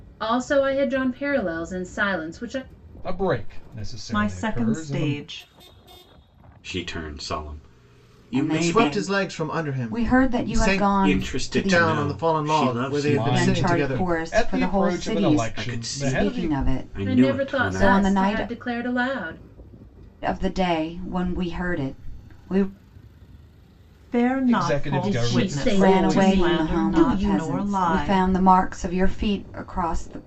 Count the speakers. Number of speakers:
6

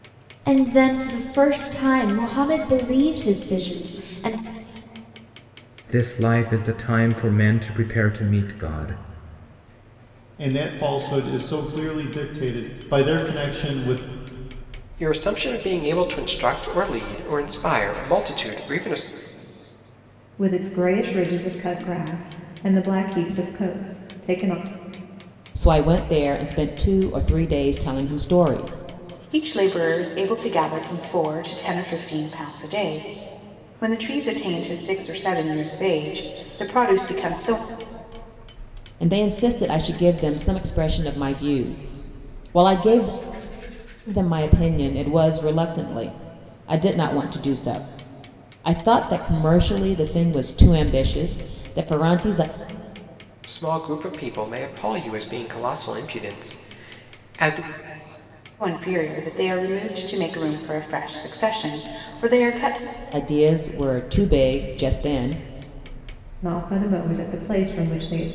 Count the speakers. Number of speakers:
7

